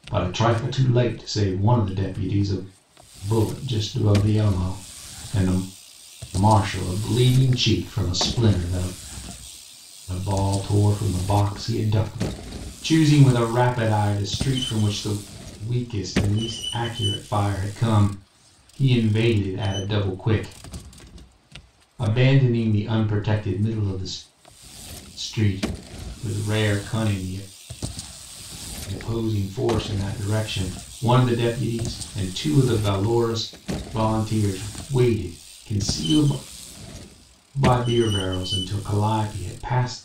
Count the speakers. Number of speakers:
1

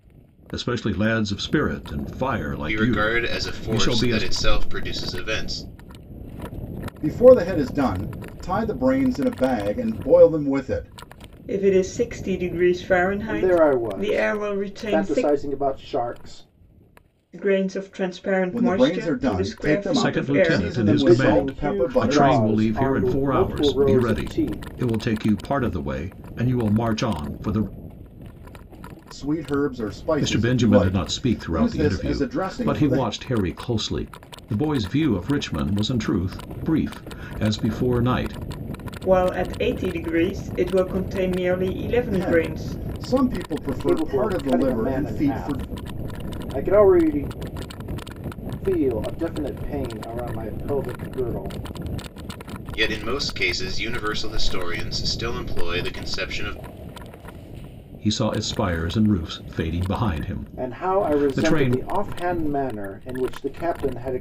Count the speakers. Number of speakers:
5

